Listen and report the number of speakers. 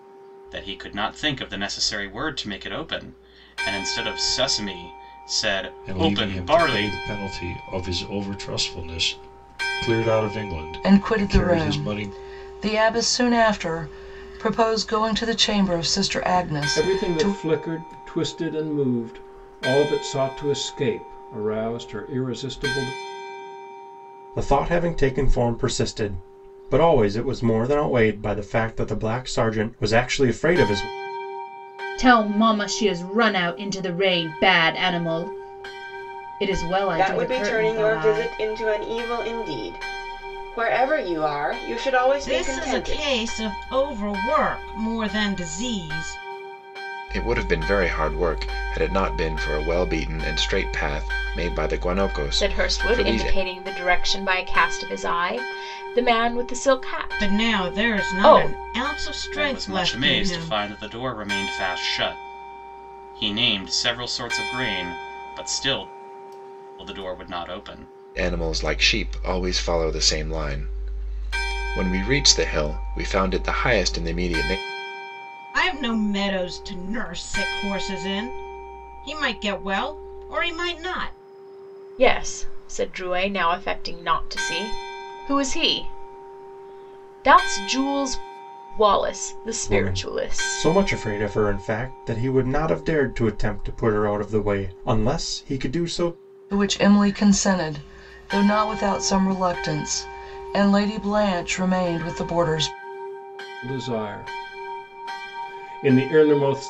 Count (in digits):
10